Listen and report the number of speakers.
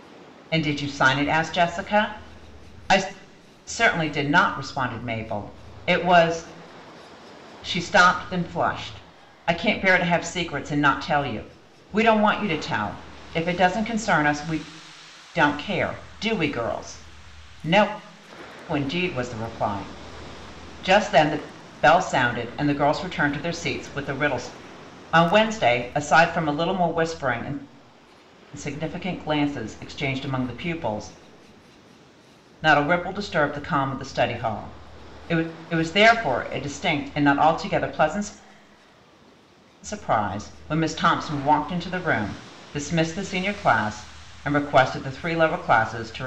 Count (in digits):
1